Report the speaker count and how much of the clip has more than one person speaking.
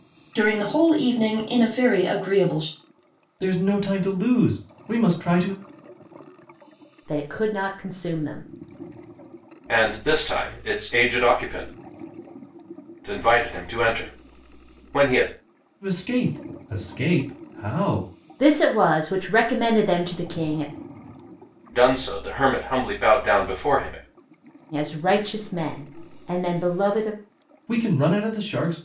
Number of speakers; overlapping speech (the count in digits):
4, no overlap